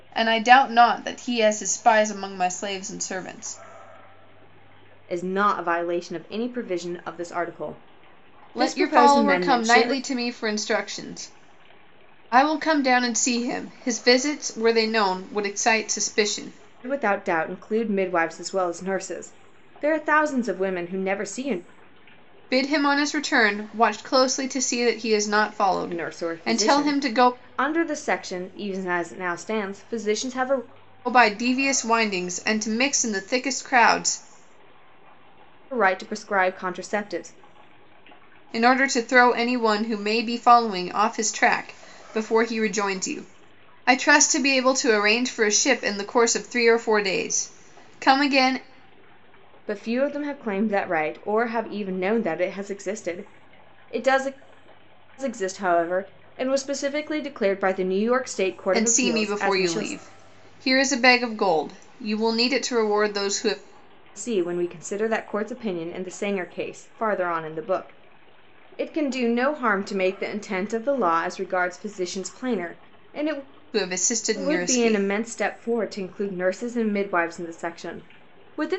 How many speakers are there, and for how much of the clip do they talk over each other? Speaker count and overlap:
2, about 6%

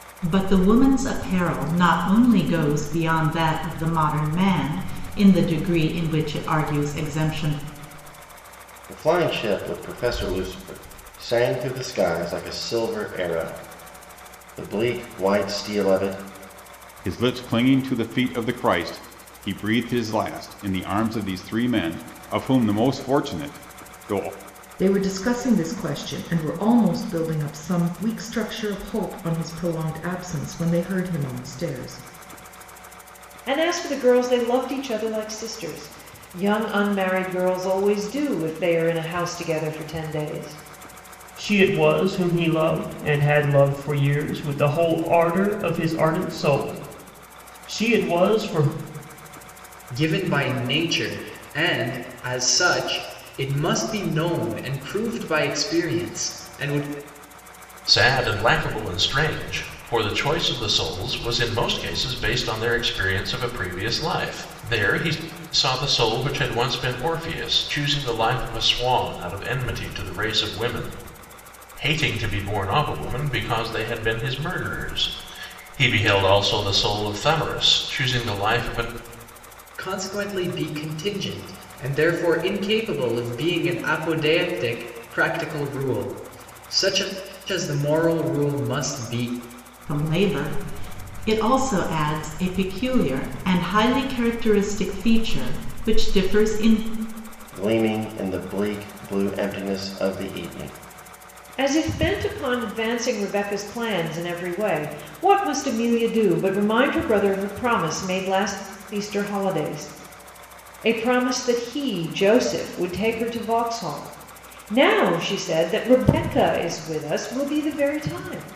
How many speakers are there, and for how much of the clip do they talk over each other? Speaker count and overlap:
8, no overlap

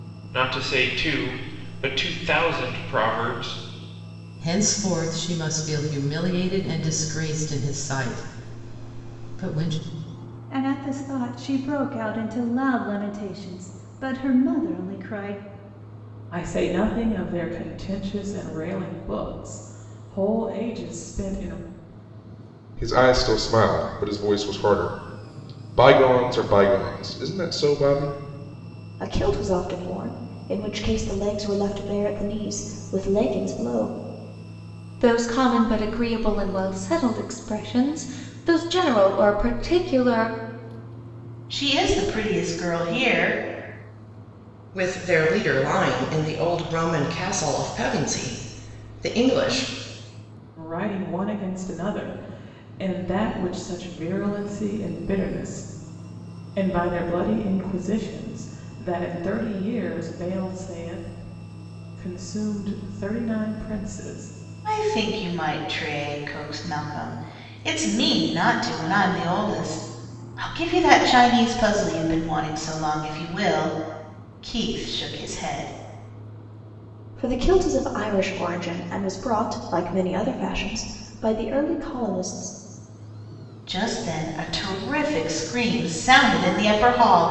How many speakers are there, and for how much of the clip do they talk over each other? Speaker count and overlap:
9, no overlap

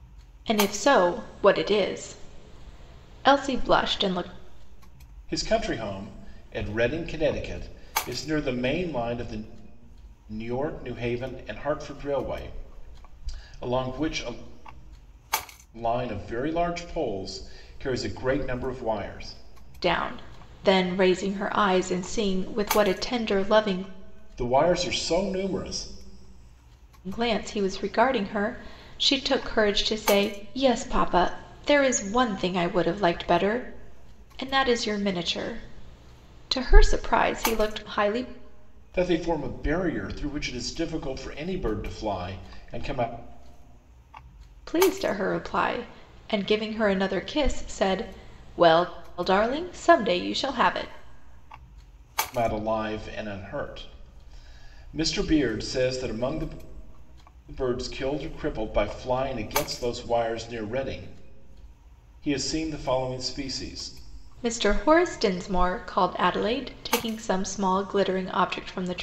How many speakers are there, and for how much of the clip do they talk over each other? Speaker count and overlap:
2, no overlap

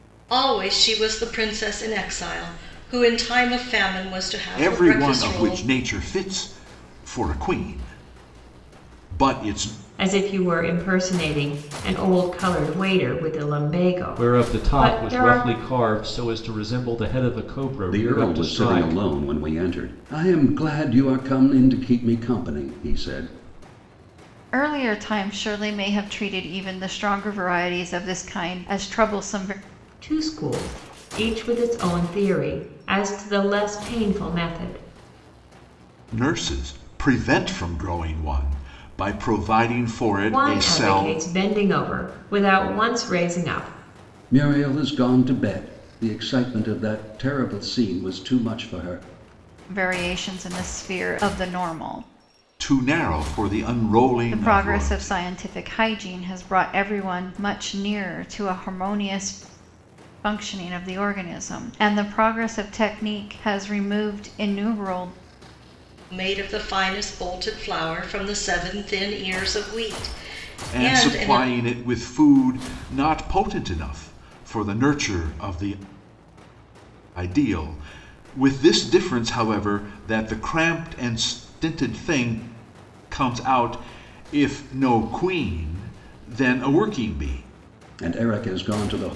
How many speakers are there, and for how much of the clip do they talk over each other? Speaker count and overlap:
6, about 7%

